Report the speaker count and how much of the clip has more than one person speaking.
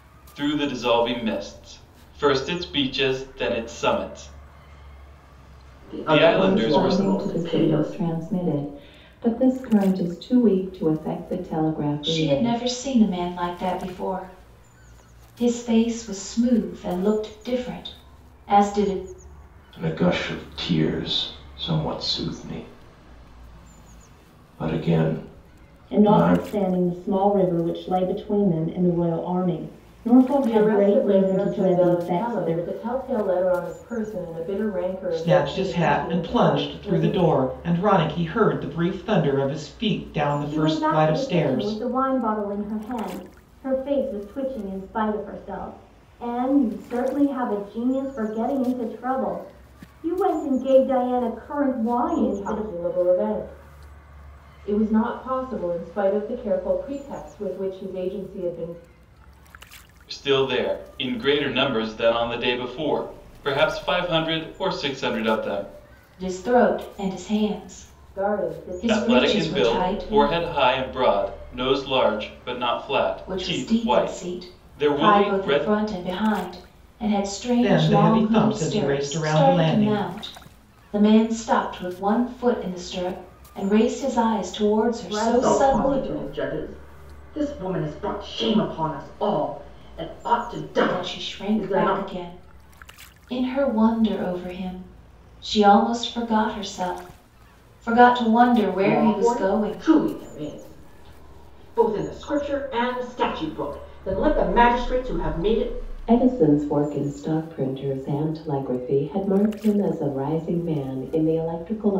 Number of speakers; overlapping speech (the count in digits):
9, about 19%